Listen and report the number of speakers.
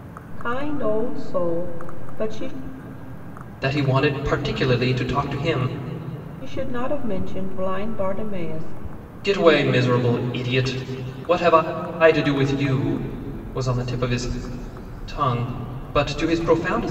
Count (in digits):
2